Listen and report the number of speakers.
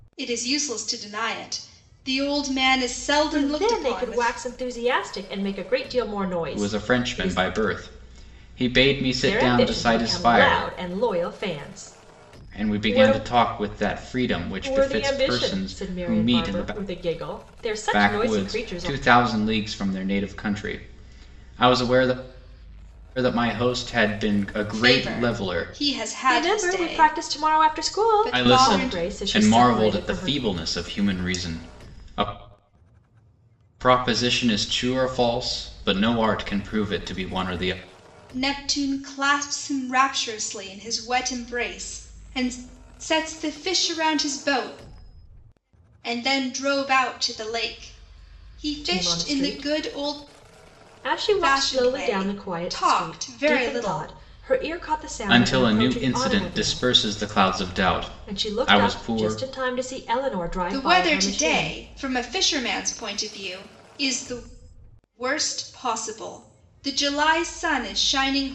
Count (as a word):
three